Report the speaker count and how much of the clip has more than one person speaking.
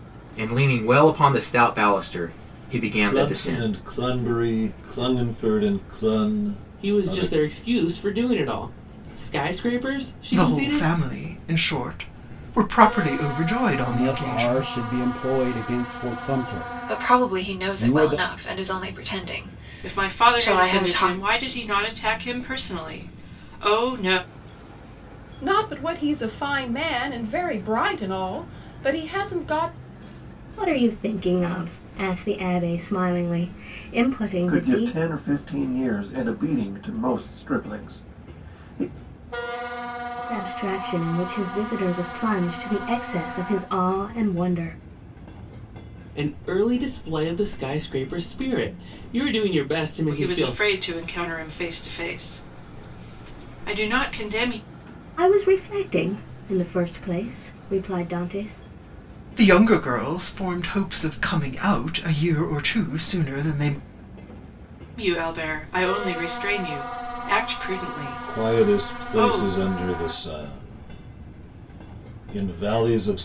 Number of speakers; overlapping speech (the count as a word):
ten, about 11%